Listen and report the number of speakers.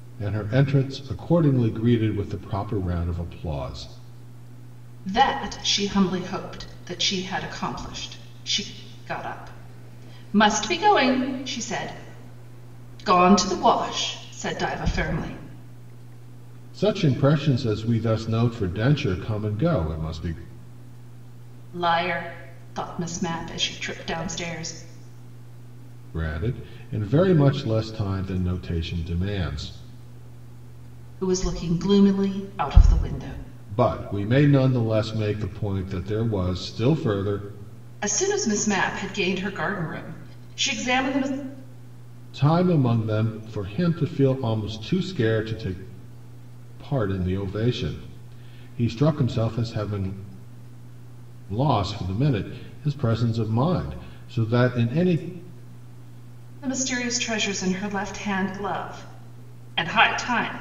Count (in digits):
2